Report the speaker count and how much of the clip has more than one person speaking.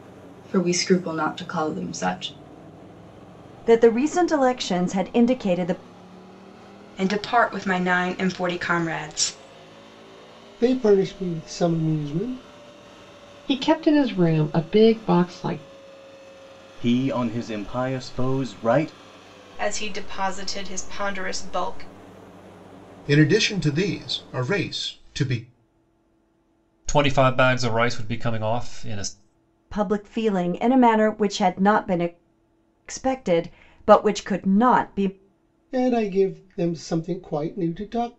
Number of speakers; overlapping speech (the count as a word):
nine, no overlap